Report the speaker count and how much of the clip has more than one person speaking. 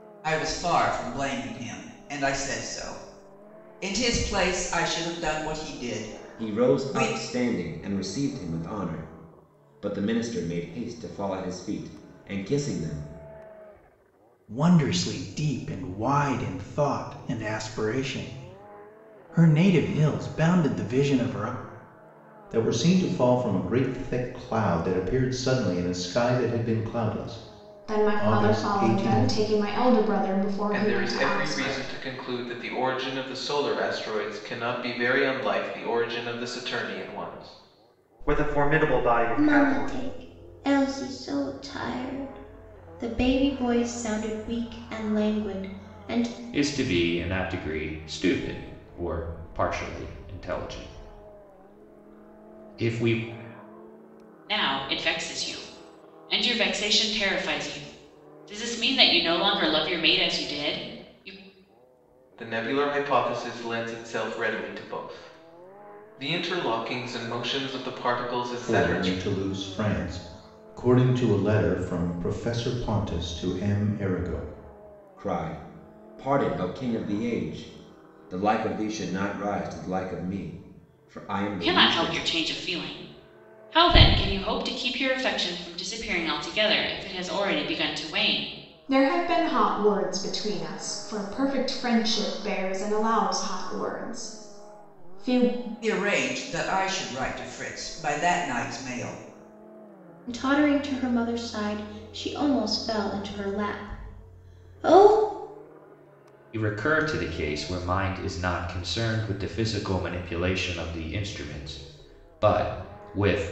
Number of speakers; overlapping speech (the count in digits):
10, about 5%